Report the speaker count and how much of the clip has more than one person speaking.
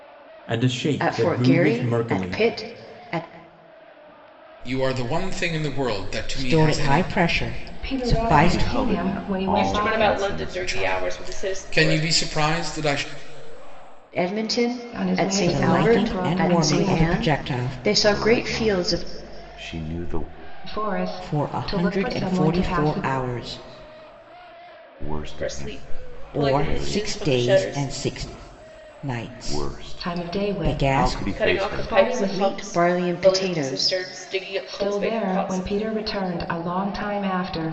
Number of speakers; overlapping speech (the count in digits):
7, about 54%